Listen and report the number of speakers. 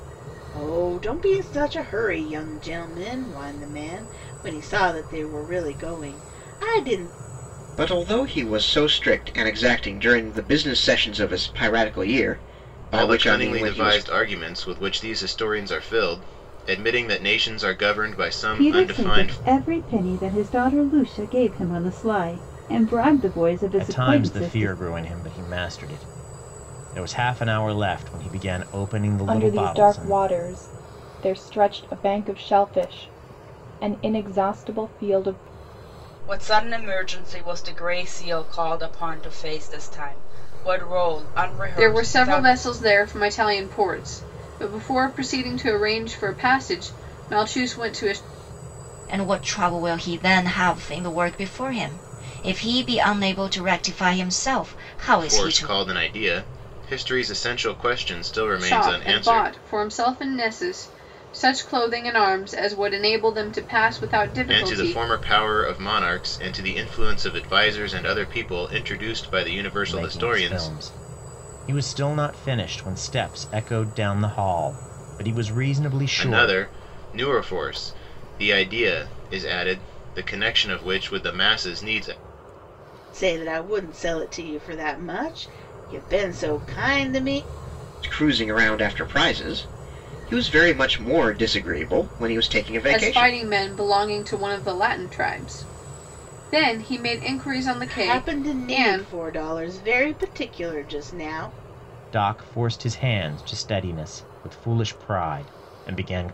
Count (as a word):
nine